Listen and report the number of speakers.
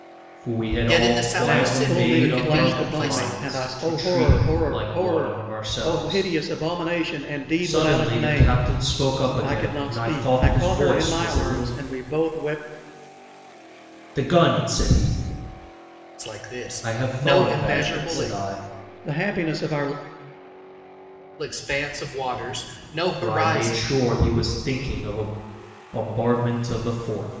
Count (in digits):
3